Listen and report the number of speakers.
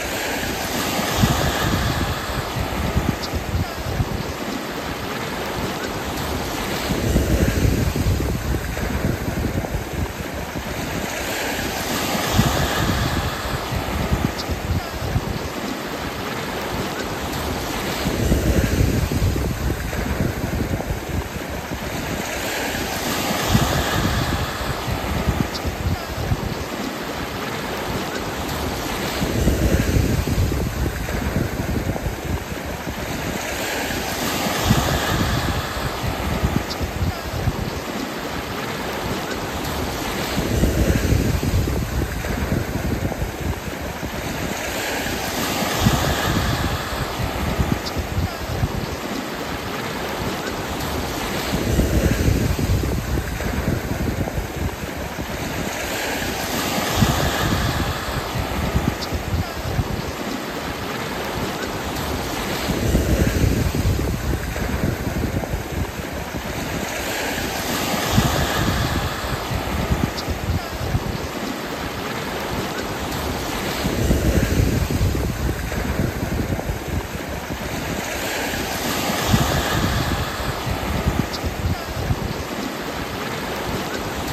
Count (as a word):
zero